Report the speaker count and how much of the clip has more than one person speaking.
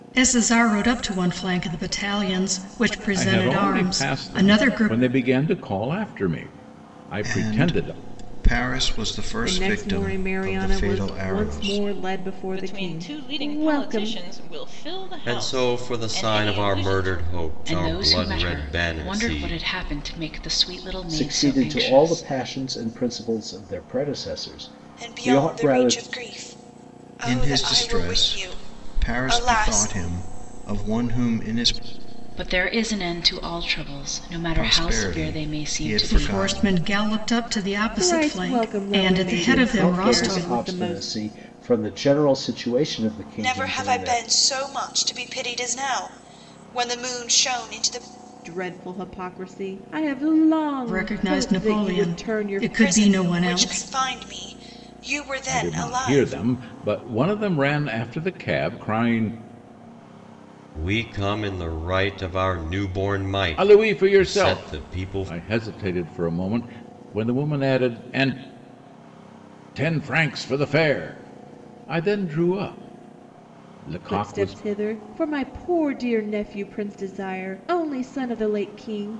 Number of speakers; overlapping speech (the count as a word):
nine, about 36%